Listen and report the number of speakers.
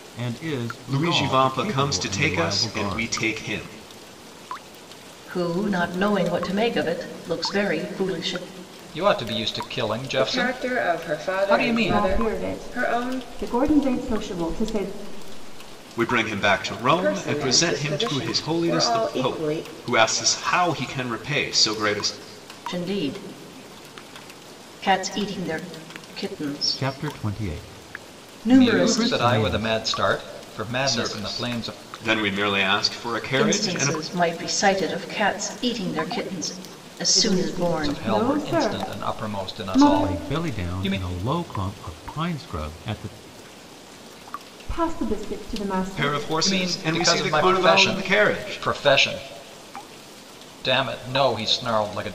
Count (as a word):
six